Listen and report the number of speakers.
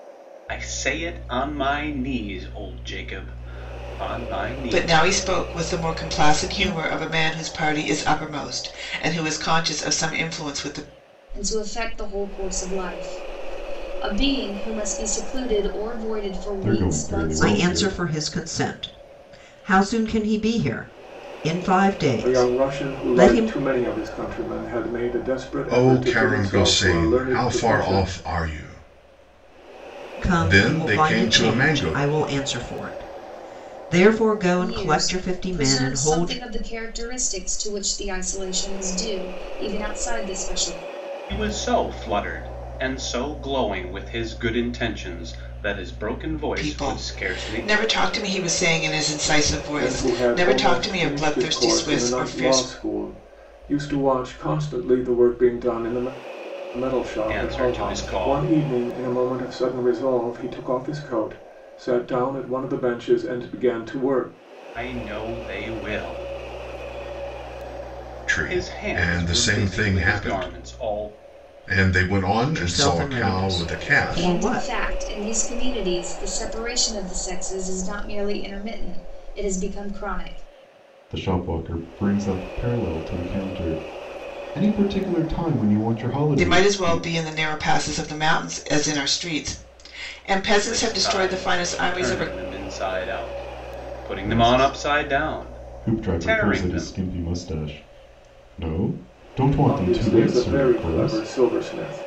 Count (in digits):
7